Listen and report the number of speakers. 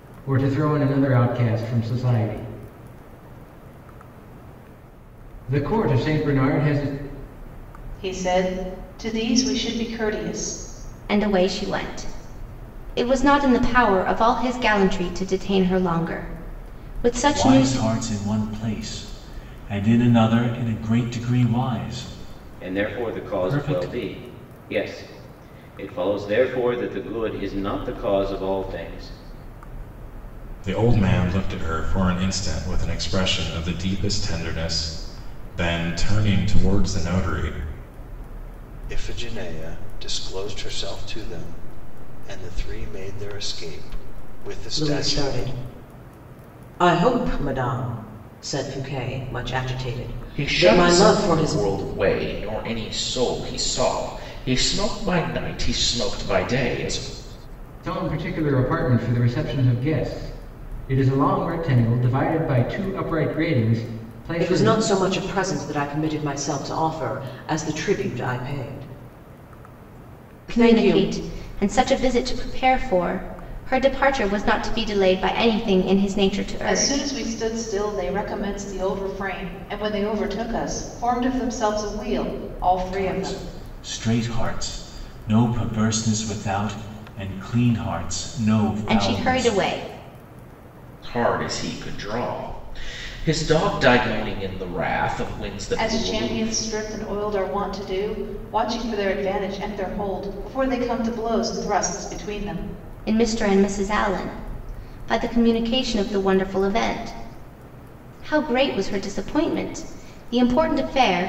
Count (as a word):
nine